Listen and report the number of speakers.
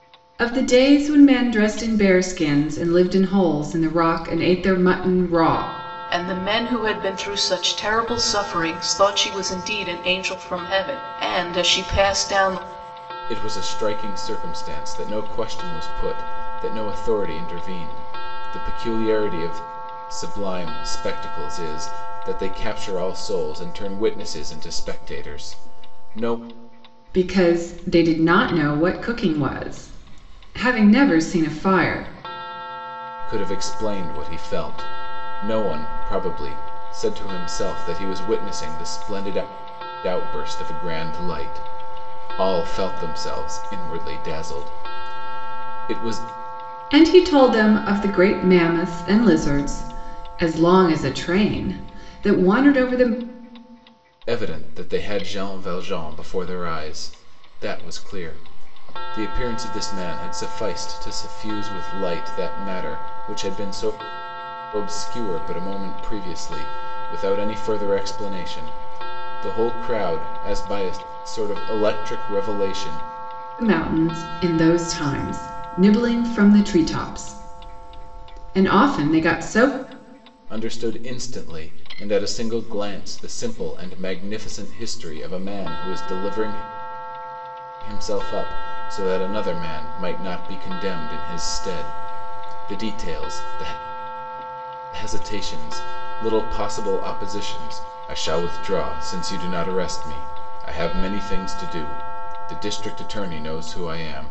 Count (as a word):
three